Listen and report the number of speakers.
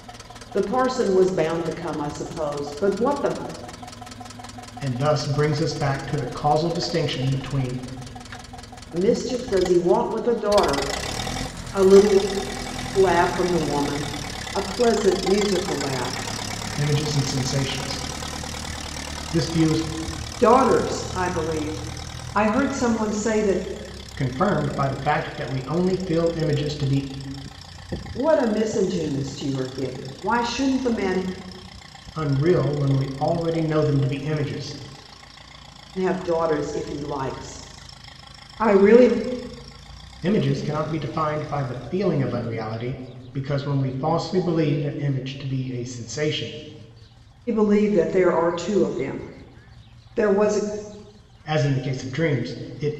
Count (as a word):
two